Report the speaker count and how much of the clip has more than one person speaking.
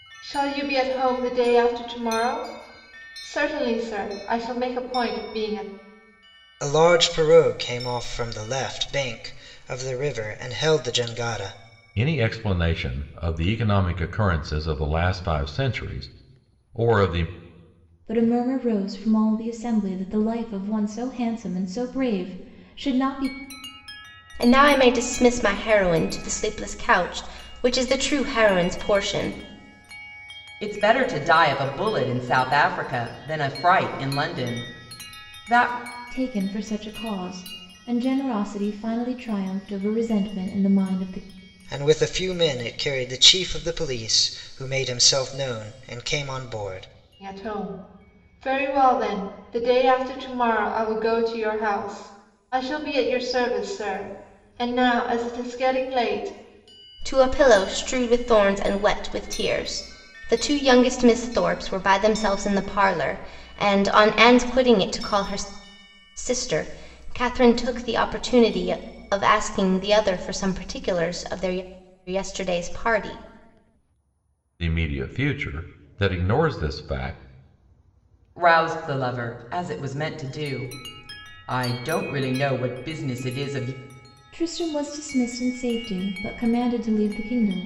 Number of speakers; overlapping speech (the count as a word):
six, no overlap